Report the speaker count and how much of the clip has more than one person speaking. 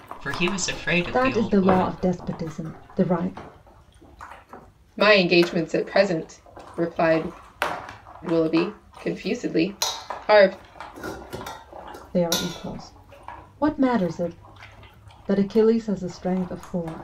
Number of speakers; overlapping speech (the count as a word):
three, about 6%